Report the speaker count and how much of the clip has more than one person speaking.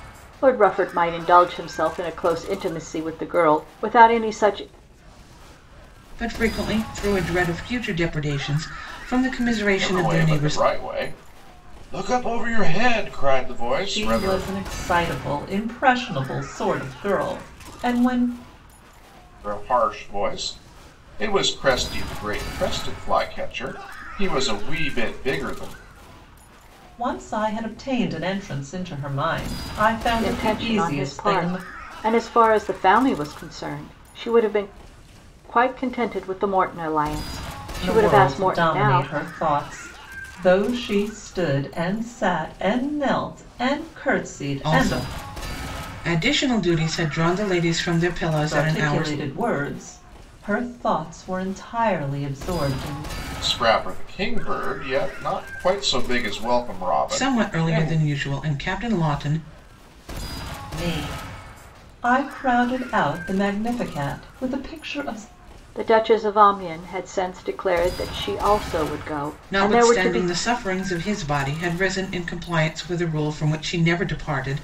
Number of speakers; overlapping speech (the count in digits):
4, about 9%